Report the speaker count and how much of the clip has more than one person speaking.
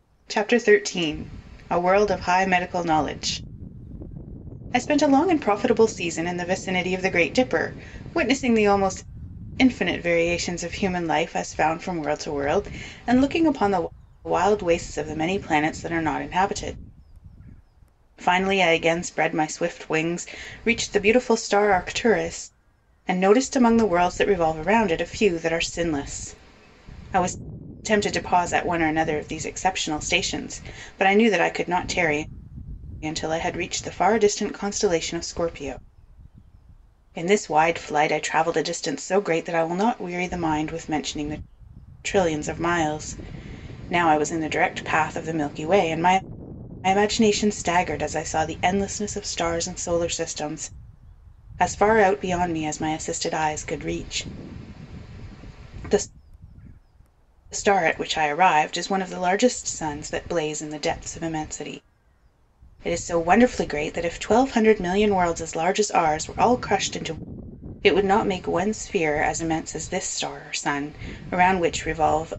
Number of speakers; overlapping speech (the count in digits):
1, no overlap